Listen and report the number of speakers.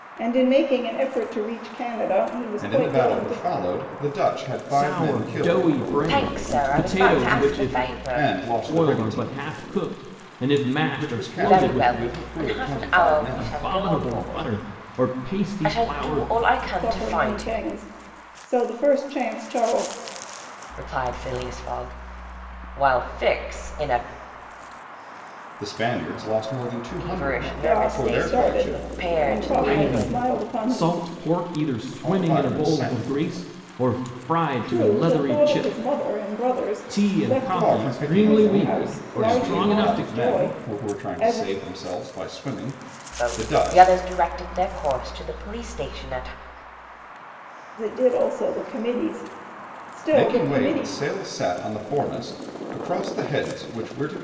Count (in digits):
4